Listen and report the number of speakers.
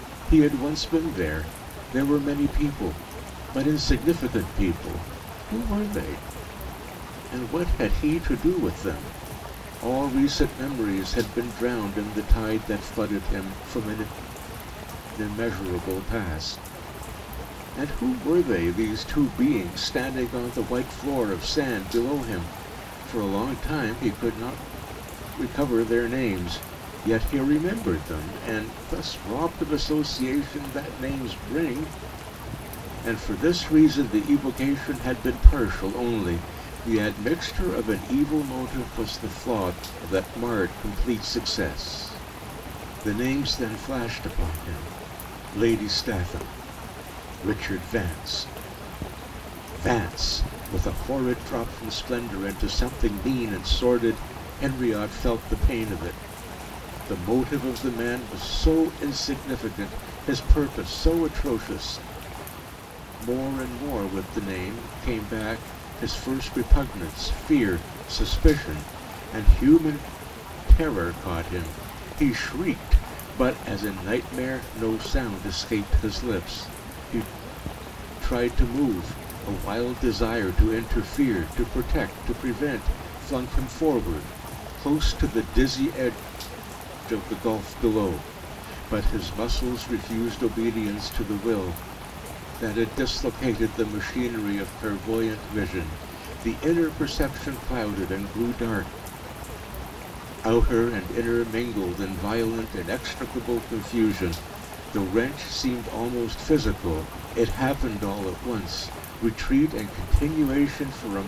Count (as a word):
one